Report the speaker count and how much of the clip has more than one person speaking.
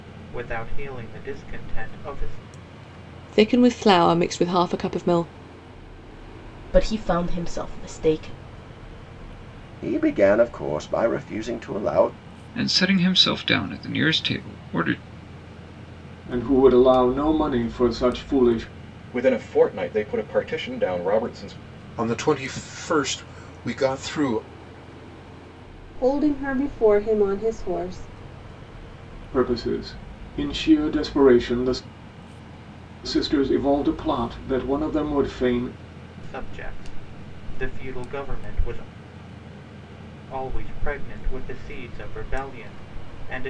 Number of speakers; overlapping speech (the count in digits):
9, no overlap